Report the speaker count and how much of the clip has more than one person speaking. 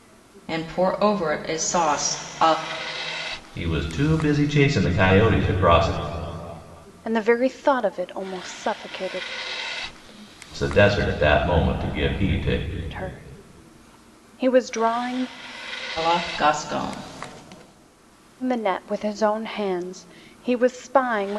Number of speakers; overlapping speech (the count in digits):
3, no overlap